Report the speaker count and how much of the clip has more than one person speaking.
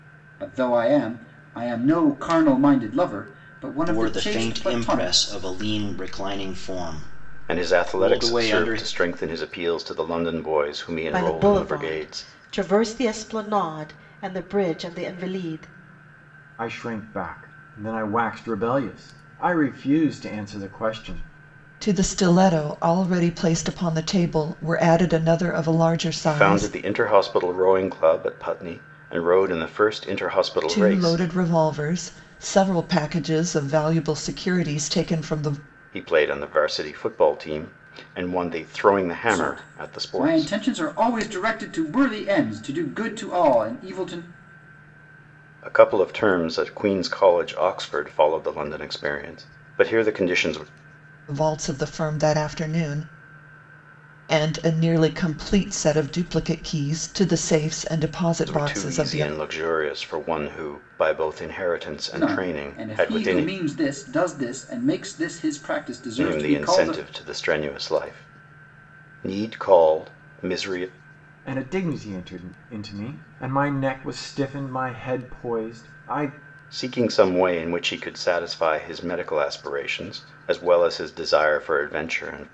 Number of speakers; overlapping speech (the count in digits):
6, about 12%